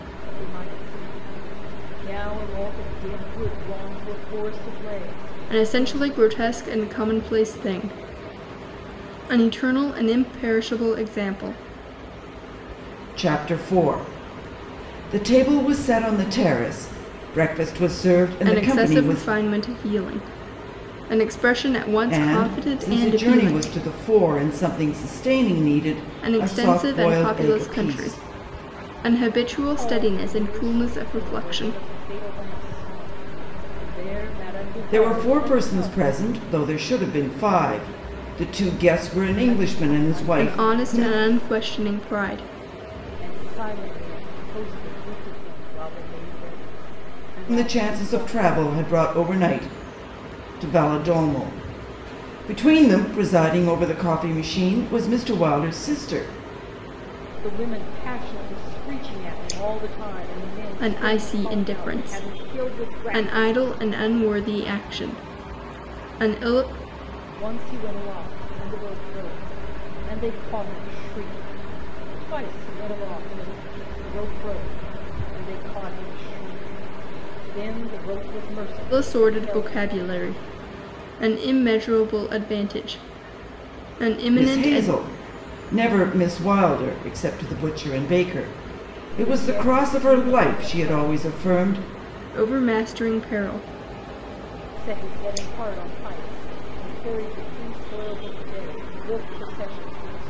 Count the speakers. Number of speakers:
3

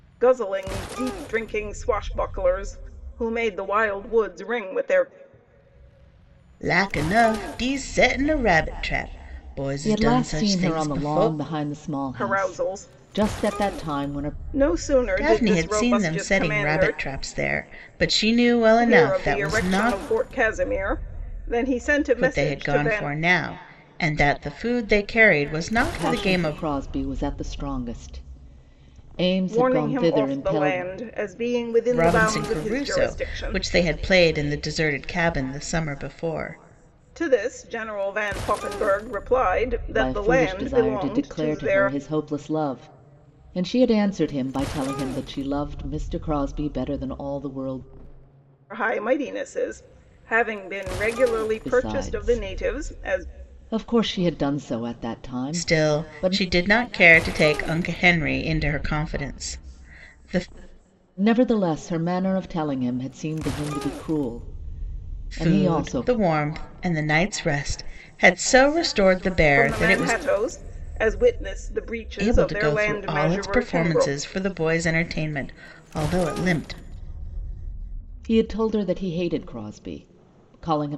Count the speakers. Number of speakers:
3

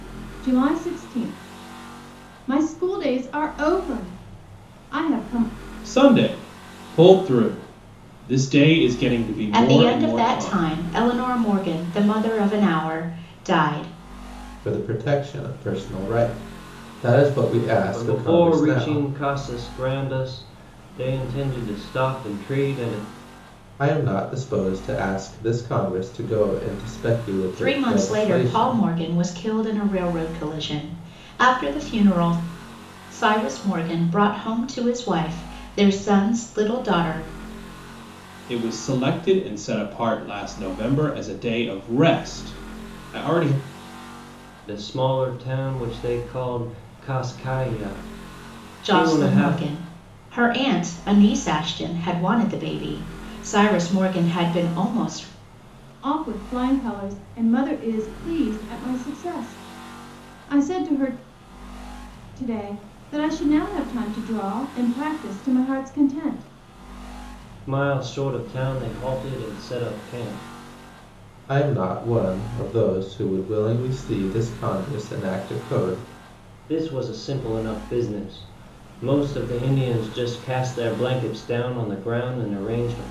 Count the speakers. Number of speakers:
5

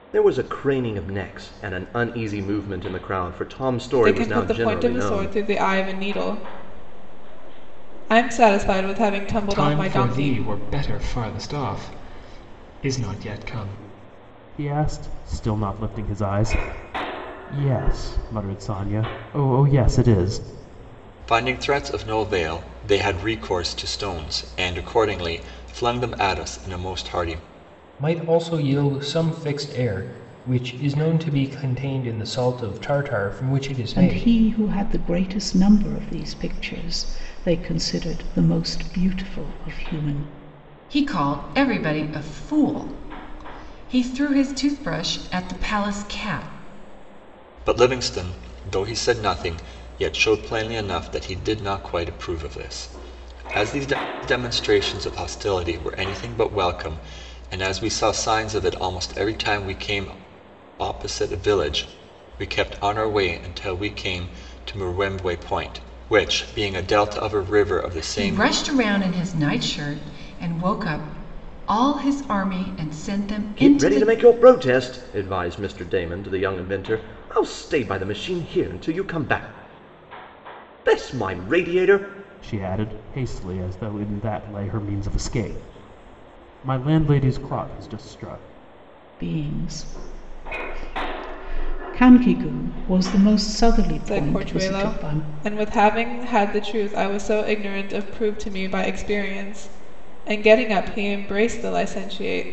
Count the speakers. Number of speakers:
8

